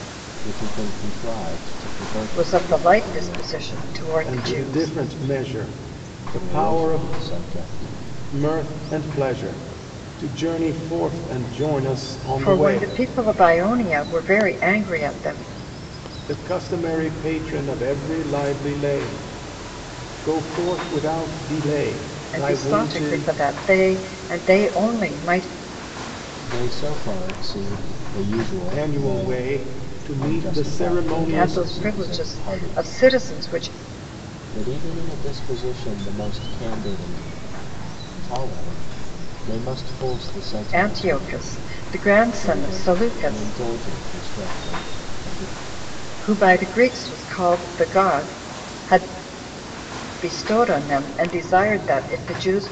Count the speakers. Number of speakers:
3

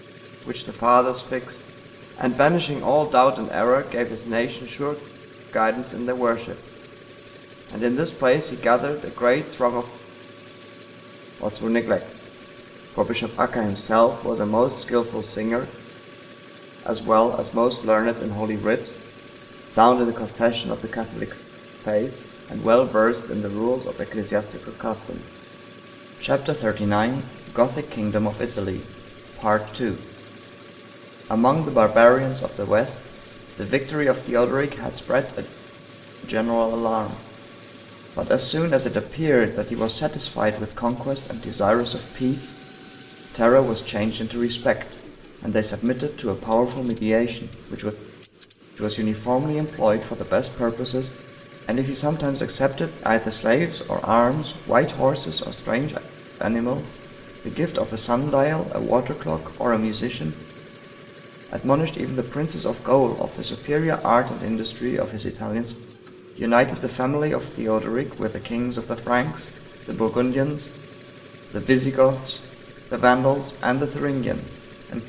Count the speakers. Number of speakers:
1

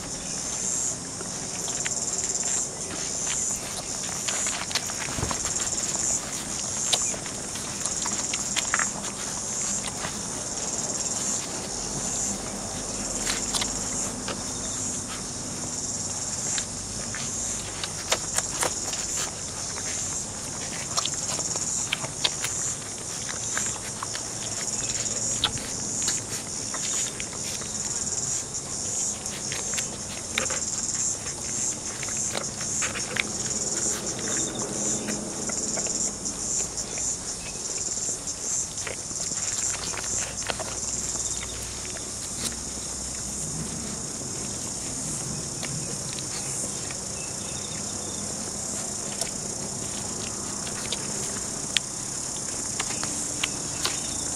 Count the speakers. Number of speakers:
0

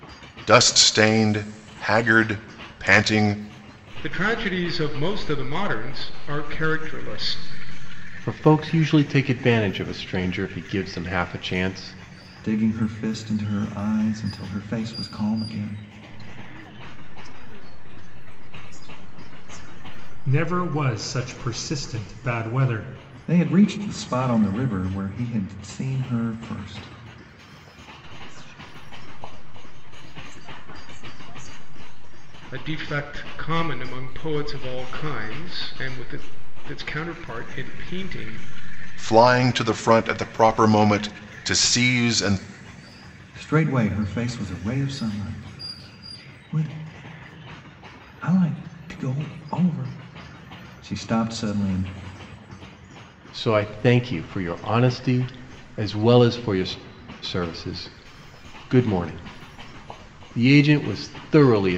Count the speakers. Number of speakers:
6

